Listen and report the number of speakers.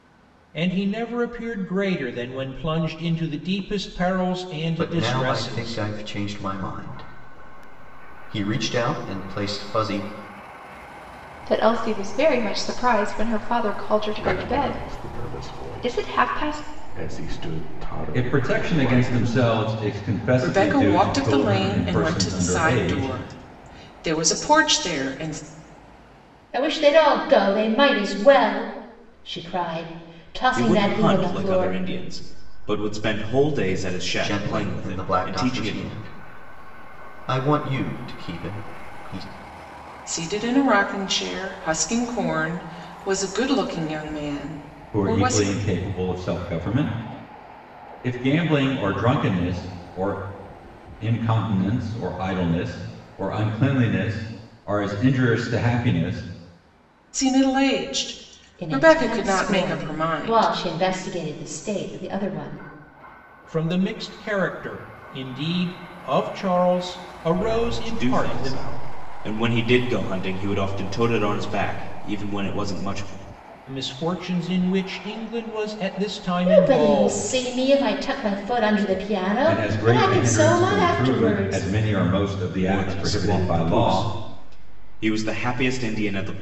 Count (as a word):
eight